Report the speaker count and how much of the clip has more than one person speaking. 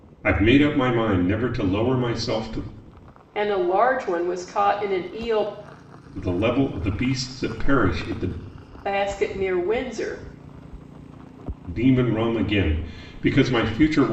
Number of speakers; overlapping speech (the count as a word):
two, no overlap